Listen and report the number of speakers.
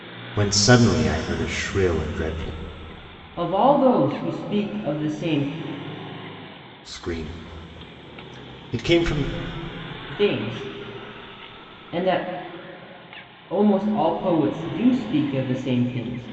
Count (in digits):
2